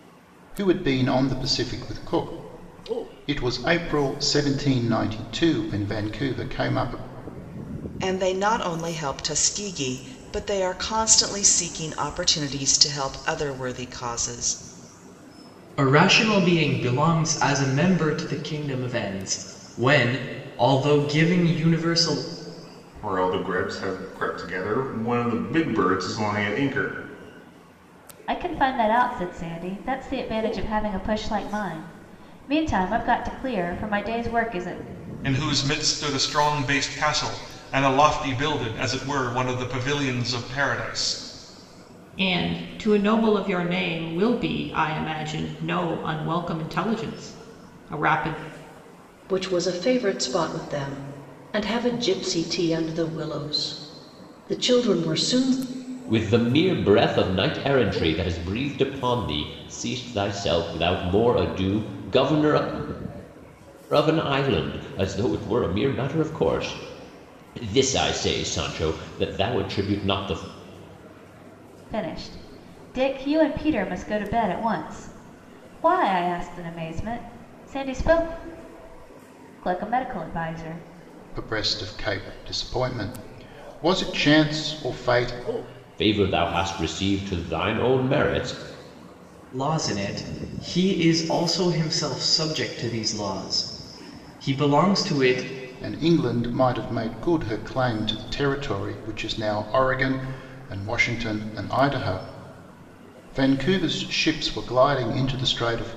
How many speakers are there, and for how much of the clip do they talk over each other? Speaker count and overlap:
9, no overlap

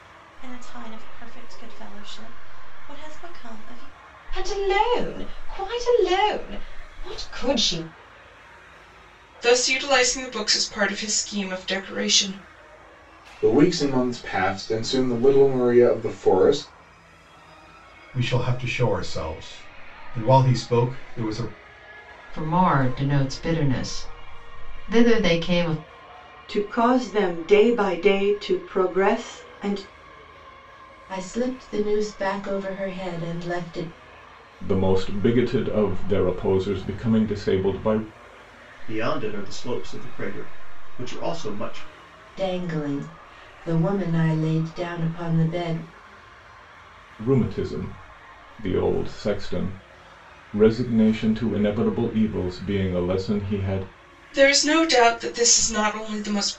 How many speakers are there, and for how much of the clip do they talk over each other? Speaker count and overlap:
10, no overlap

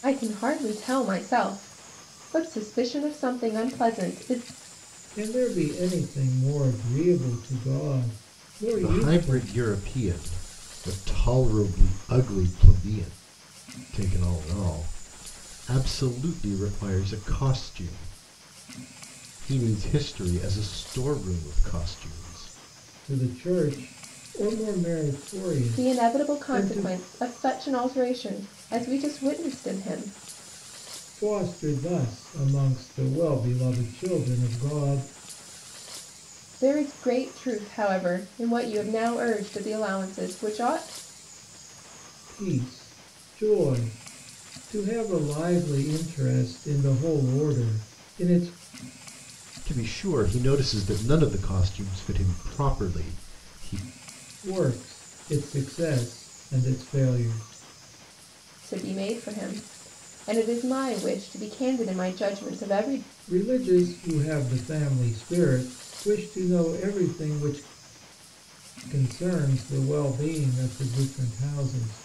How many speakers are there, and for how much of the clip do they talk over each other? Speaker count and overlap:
3, about 3%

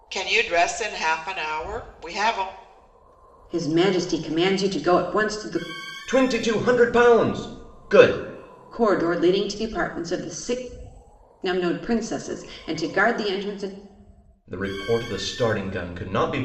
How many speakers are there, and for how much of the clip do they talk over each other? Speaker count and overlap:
3, no overlap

